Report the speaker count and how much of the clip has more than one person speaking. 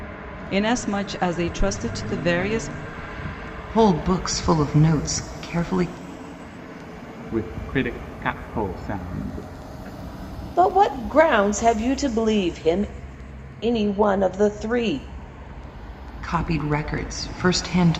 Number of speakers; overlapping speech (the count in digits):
4, no overlap